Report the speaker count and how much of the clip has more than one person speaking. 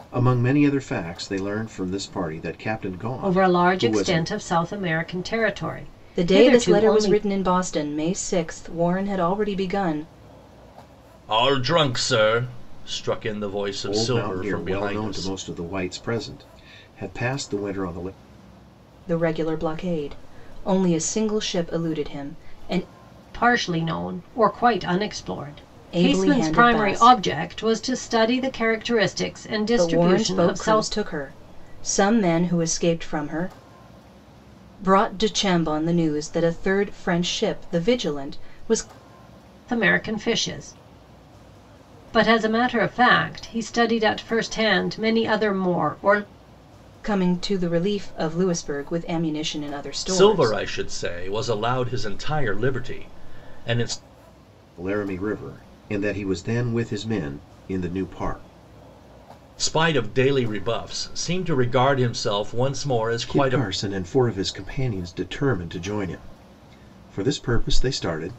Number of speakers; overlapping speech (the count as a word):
four, about 11%